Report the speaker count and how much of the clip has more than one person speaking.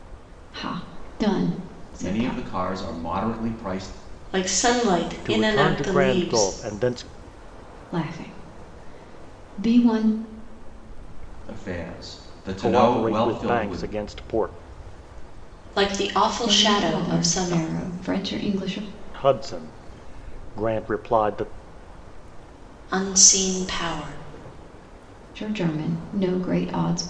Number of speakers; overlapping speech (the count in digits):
4, about 17%